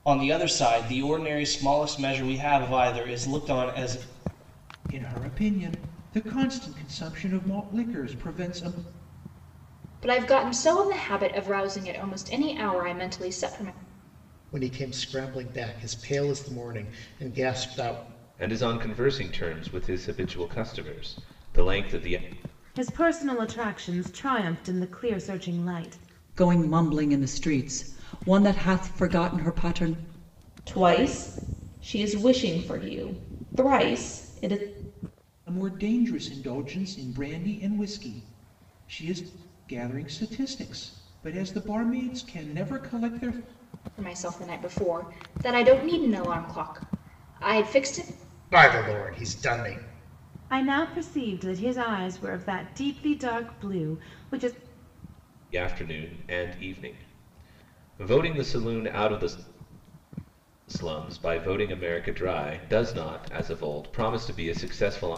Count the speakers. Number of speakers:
8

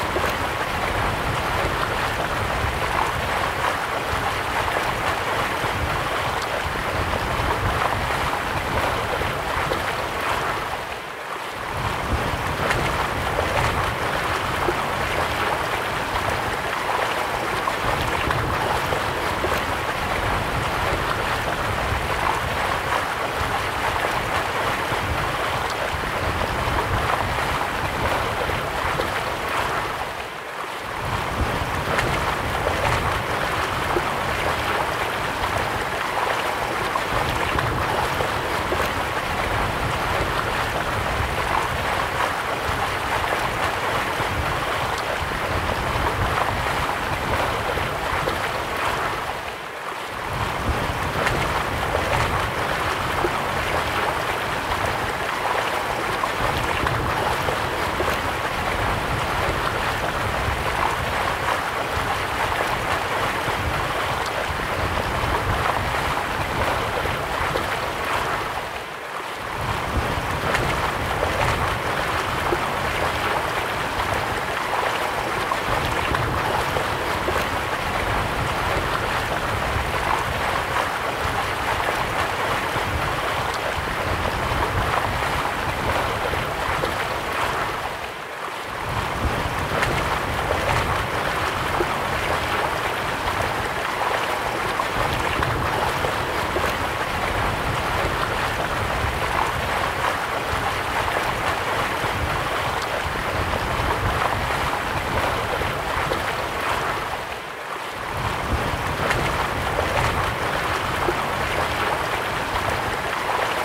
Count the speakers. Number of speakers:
0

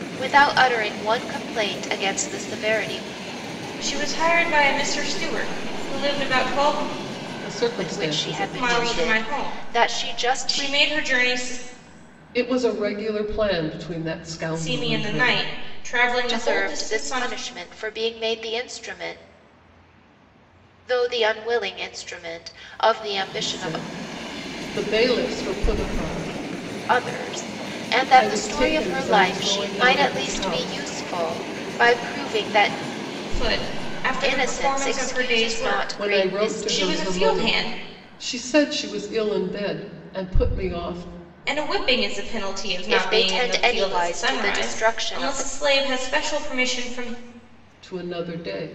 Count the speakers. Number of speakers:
3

